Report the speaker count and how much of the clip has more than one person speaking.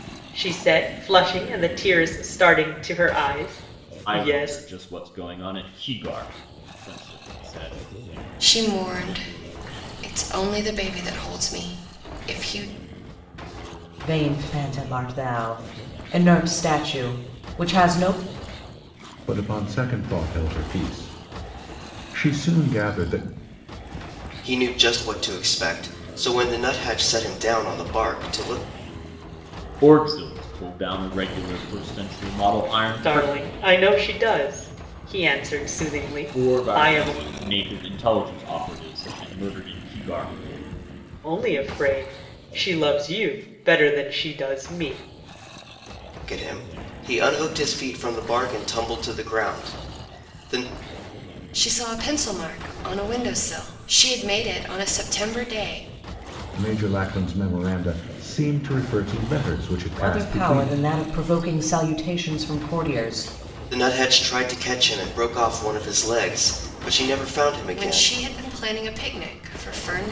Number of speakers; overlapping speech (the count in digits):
6, about 5%